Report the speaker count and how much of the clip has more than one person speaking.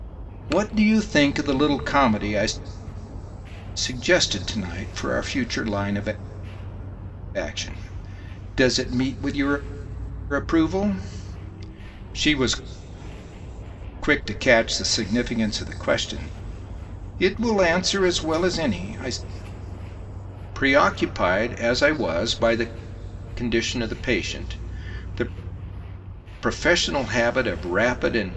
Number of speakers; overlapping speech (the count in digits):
1, no overlap